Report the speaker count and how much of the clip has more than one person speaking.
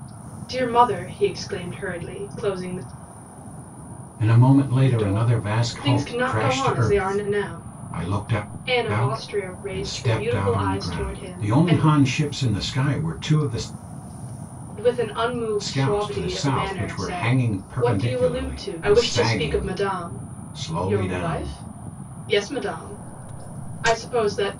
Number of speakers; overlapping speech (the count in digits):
2, about 48%